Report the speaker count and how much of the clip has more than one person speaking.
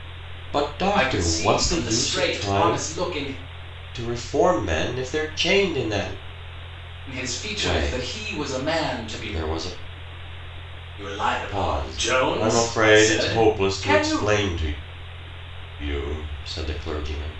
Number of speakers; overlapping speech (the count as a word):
two, about 36%